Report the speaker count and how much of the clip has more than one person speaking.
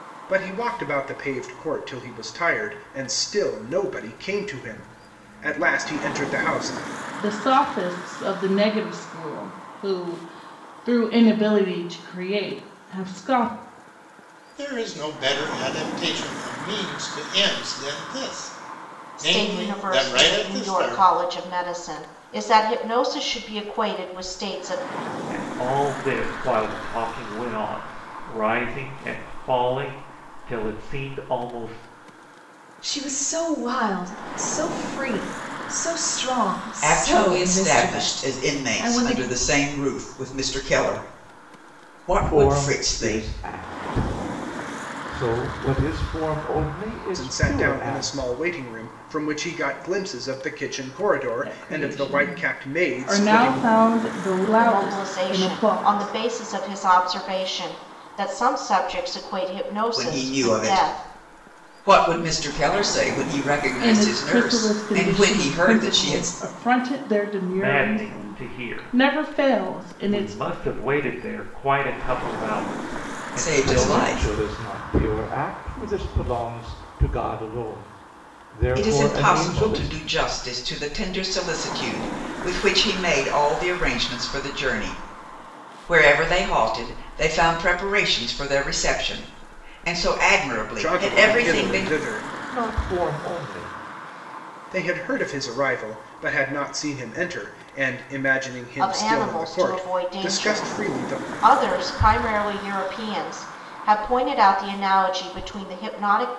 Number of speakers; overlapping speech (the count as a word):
eight, about 22%